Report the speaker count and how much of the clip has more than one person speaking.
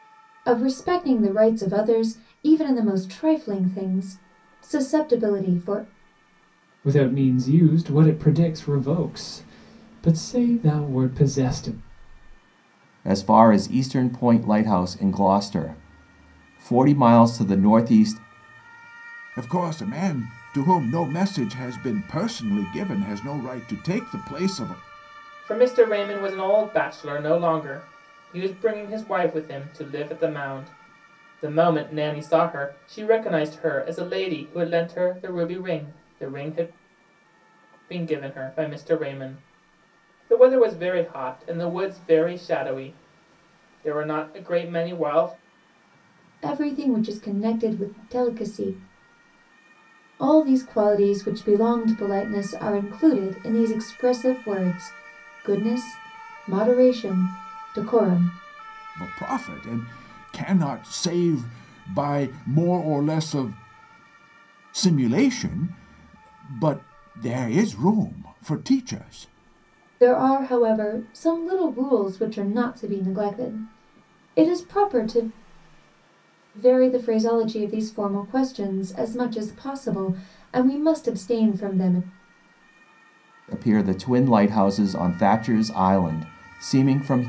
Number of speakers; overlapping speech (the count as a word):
five, no overlap